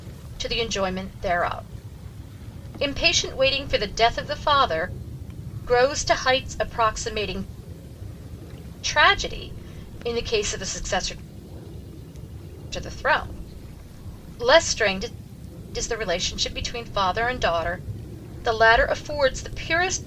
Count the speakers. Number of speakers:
1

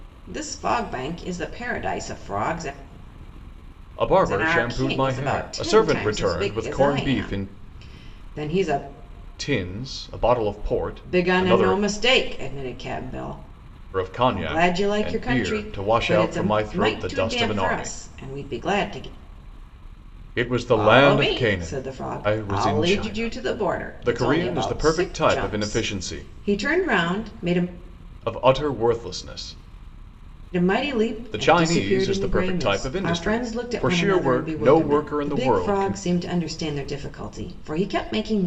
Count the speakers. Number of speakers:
2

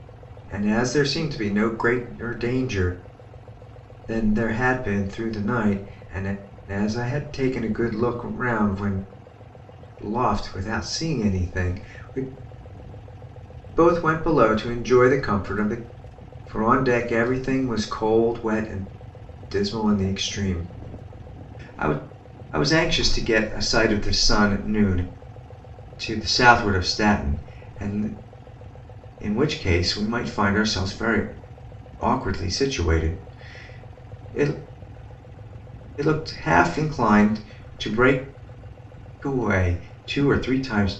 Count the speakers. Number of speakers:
1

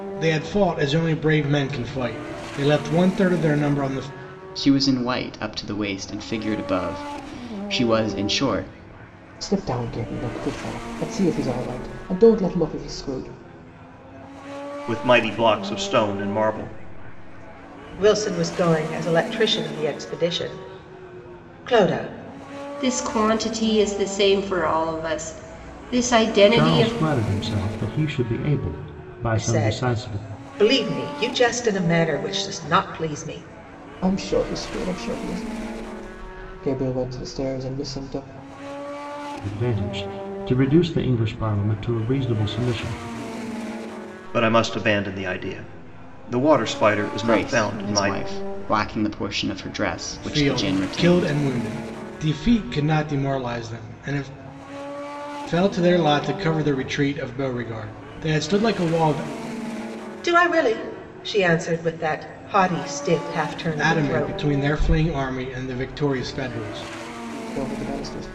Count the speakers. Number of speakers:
7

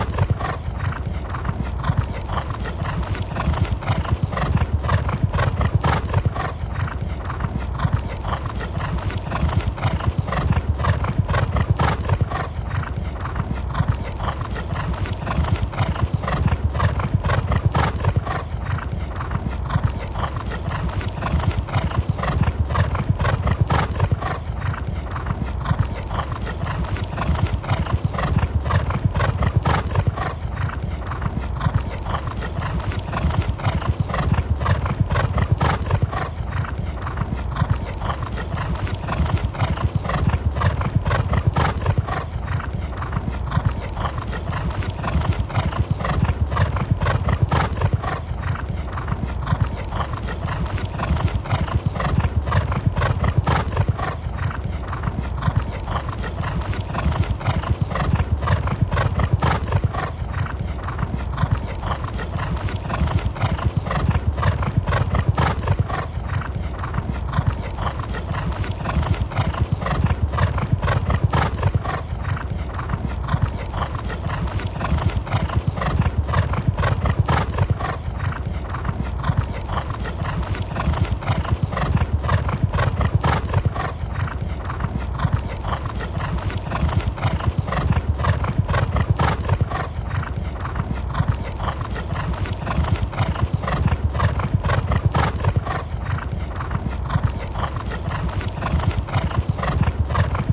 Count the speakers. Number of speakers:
0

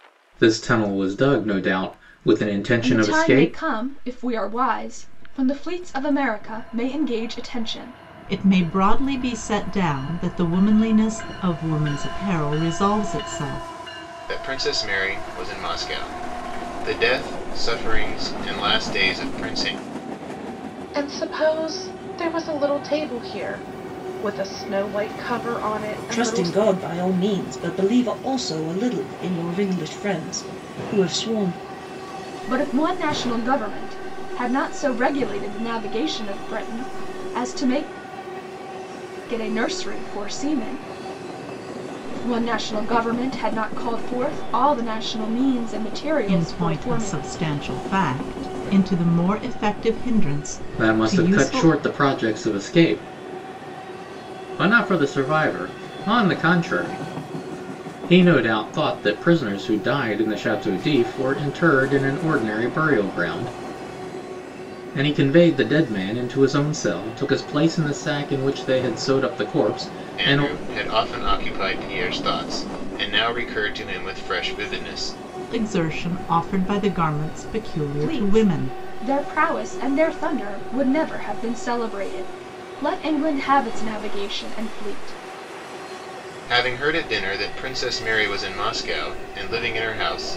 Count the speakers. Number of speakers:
6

